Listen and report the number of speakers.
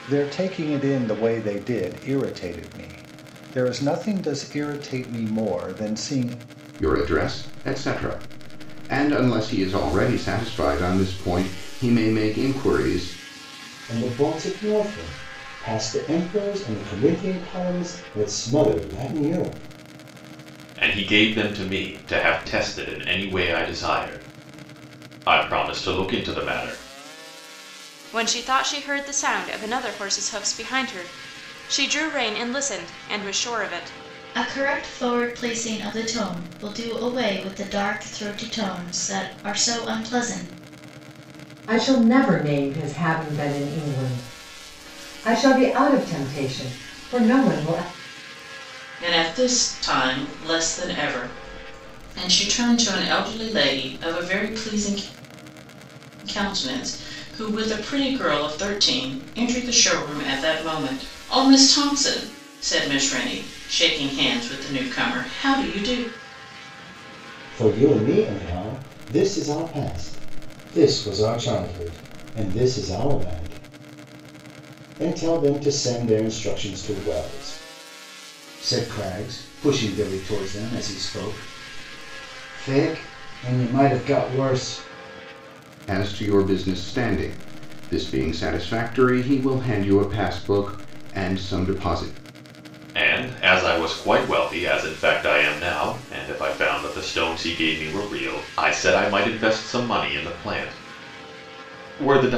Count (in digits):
8